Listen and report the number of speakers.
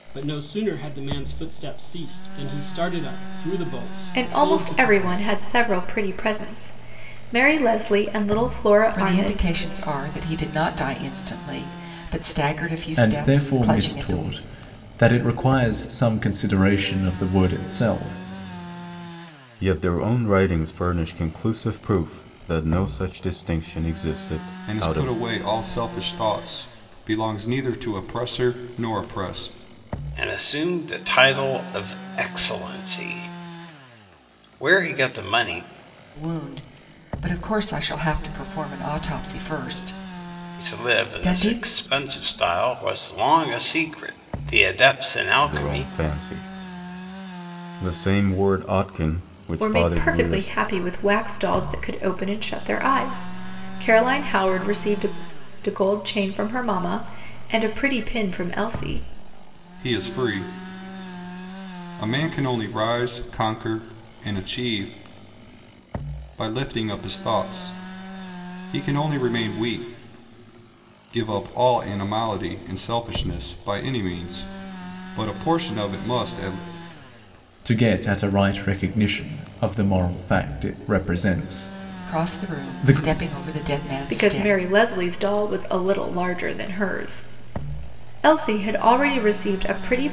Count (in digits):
7